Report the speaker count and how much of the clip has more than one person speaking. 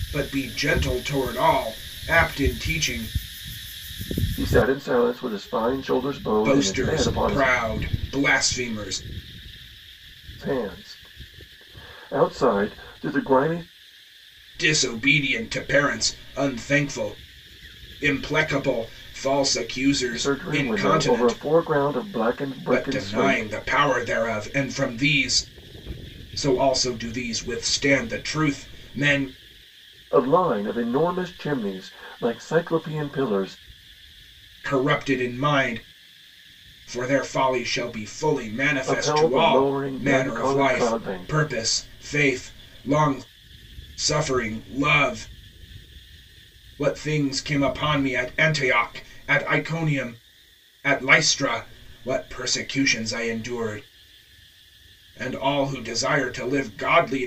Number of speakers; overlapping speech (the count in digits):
2, about 10%